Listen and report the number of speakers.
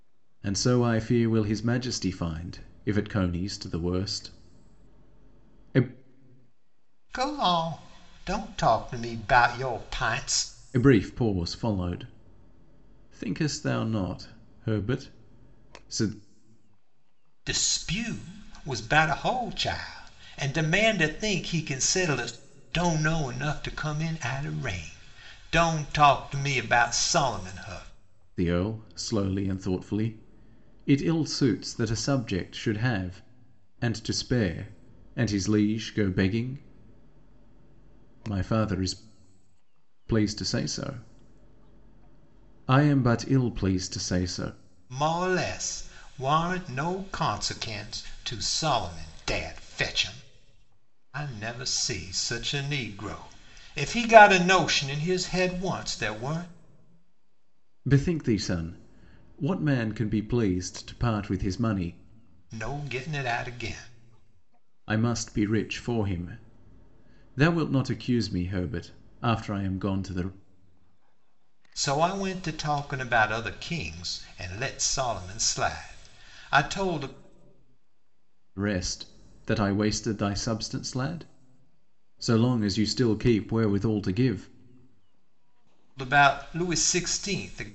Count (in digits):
2